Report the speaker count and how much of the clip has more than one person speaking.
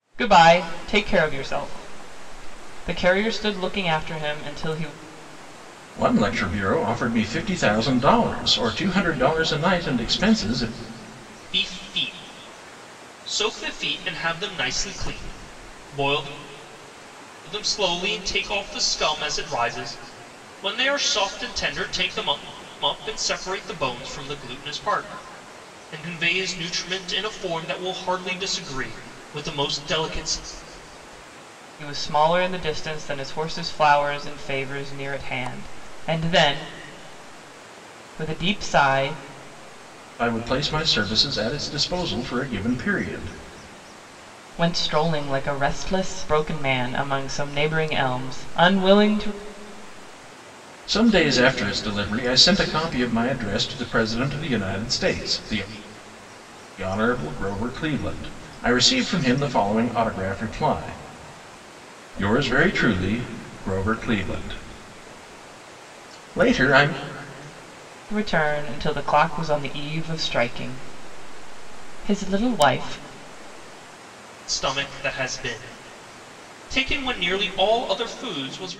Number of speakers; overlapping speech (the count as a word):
three, no overlap